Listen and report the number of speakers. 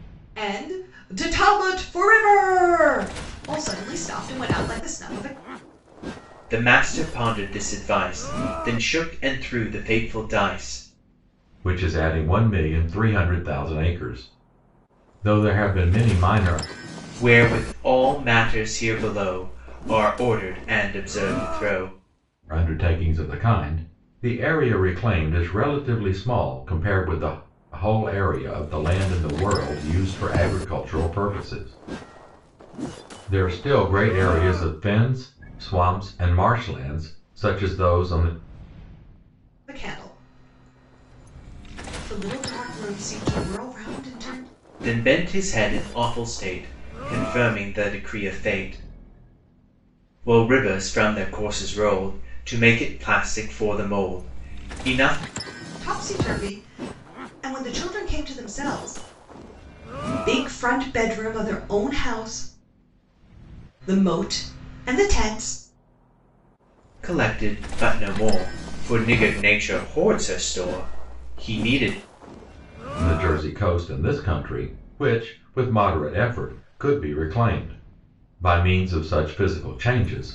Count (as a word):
three